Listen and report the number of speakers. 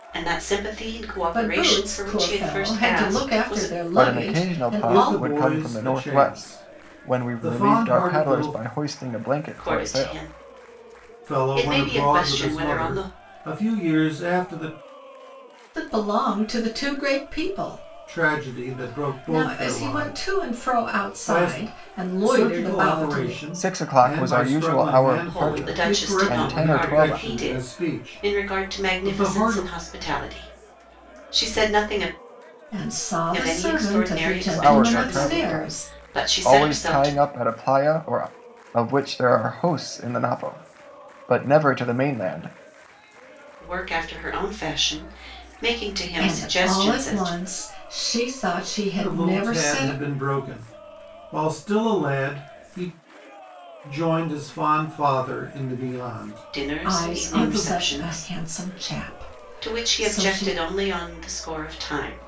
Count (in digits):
4